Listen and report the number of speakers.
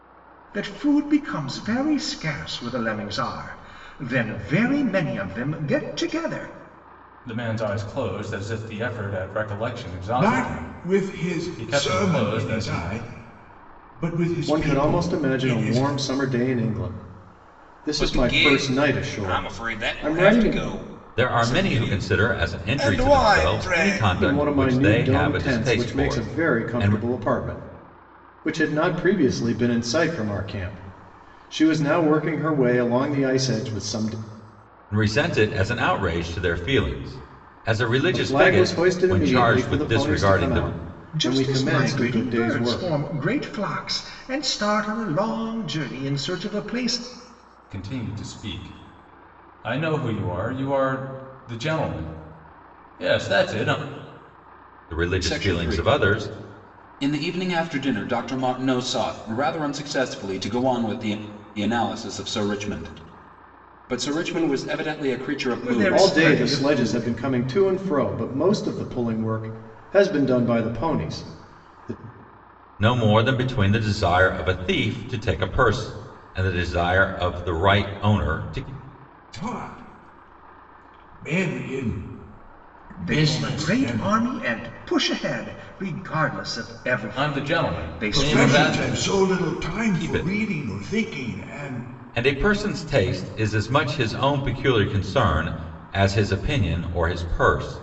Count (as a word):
six